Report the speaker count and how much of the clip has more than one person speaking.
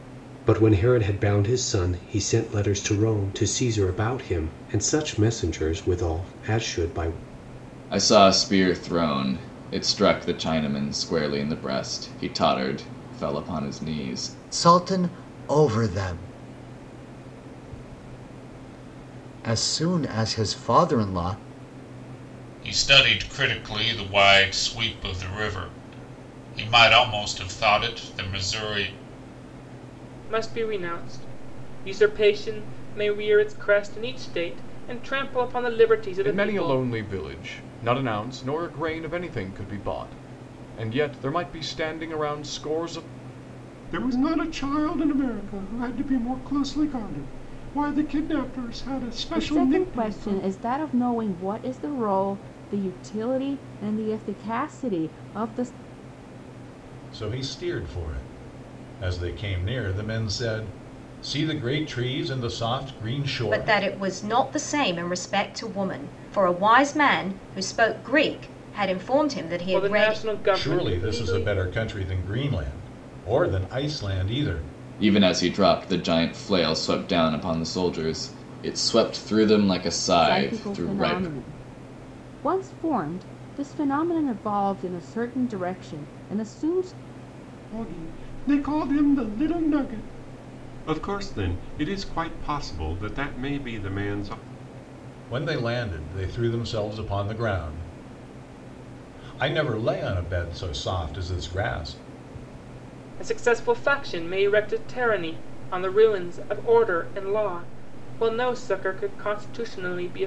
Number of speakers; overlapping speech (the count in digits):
10, about 4%